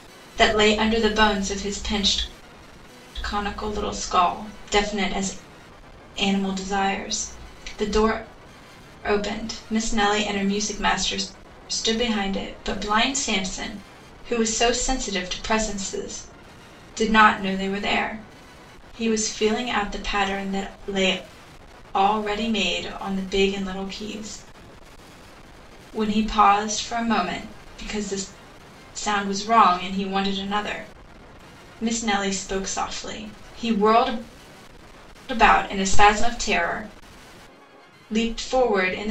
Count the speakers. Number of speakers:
one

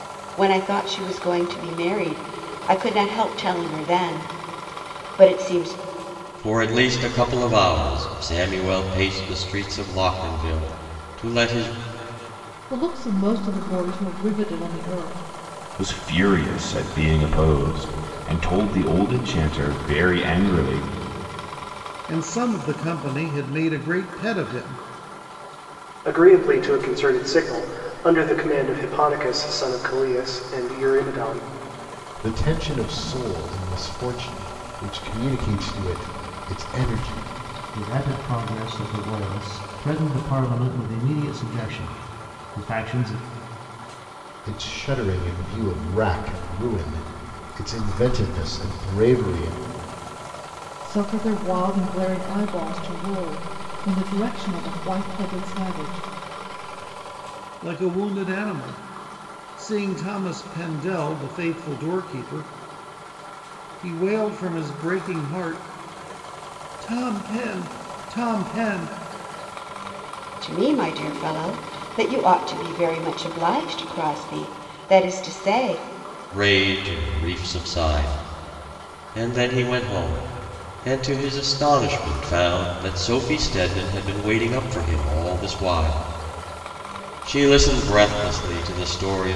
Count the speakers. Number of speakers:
eight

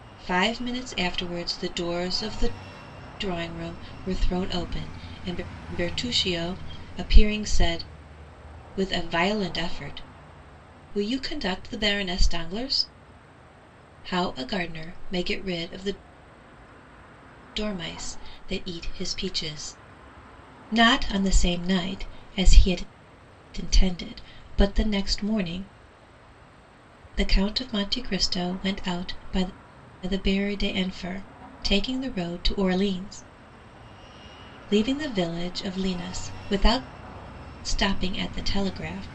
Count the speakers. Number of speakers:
one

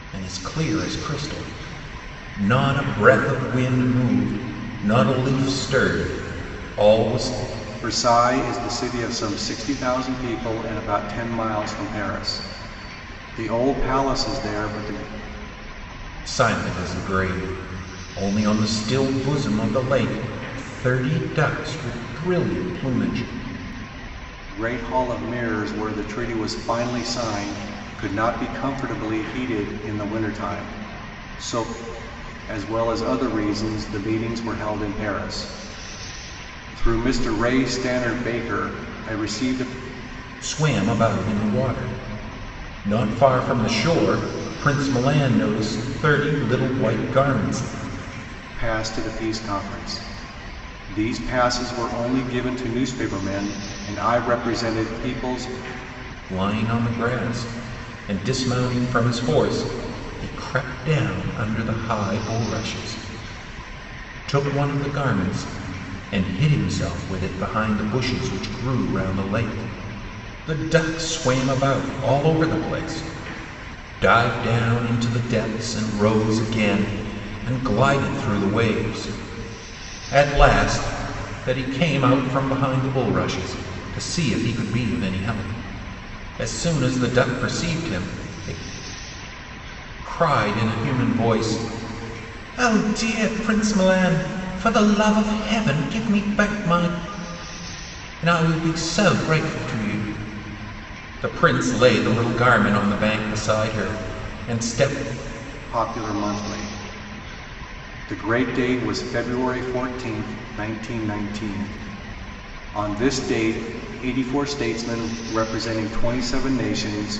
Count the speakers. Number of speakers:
two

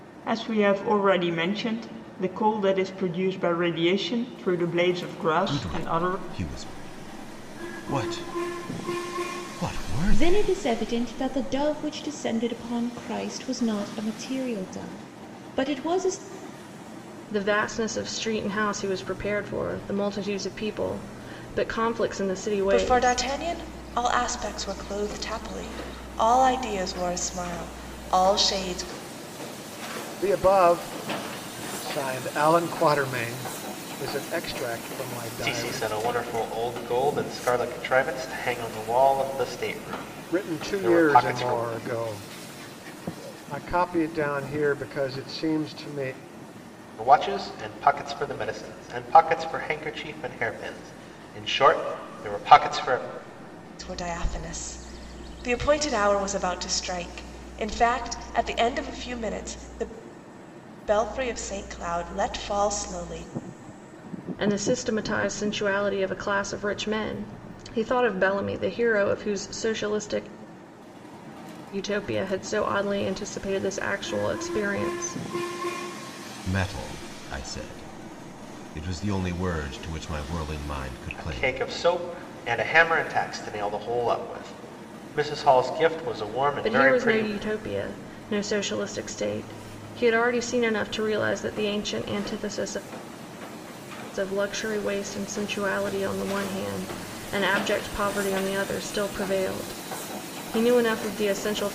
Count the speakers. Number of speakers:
seven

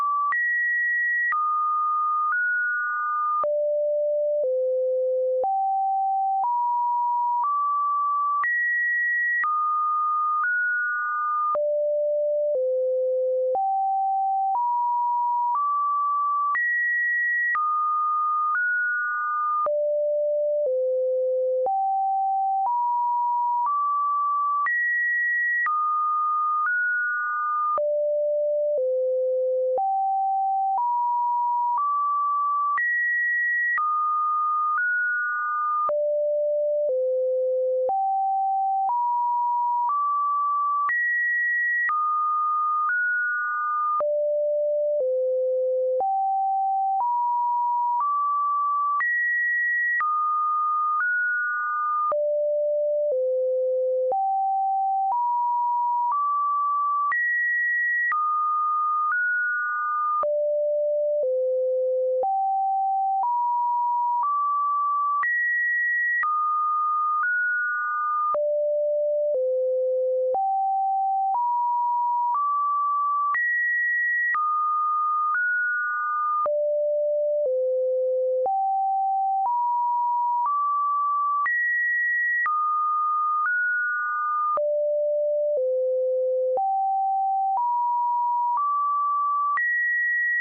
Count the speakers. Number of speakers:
zero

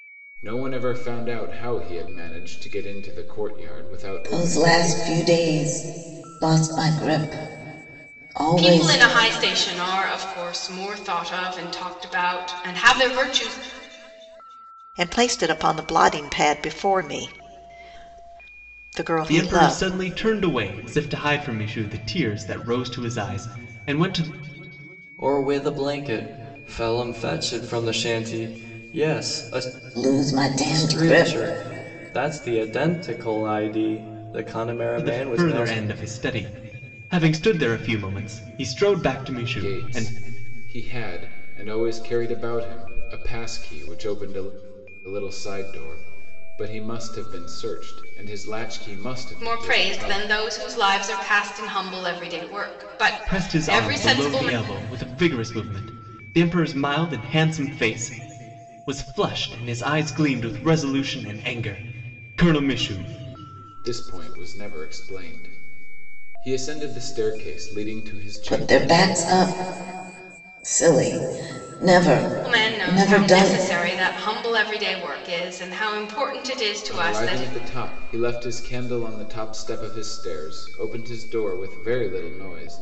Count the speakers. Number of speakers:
six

